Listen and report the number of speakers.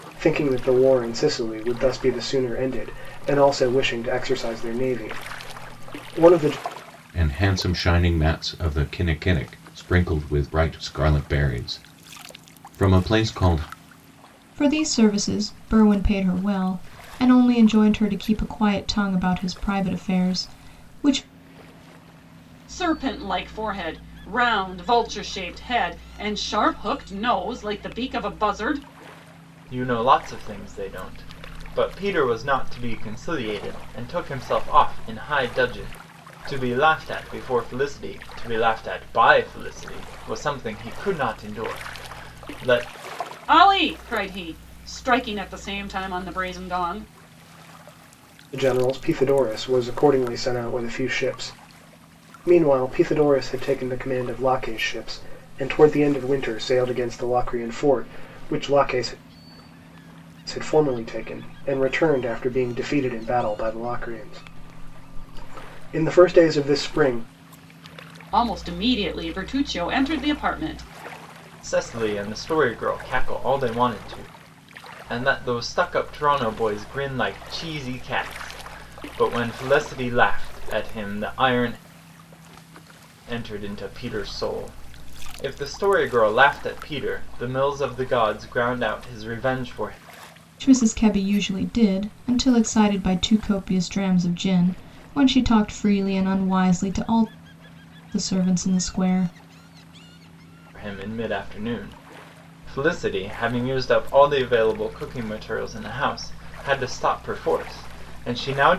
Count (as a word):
five